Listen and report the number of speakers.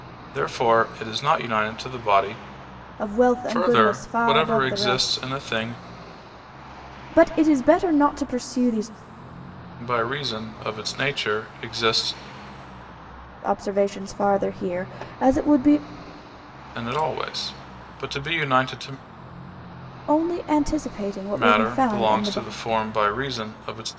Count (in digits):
2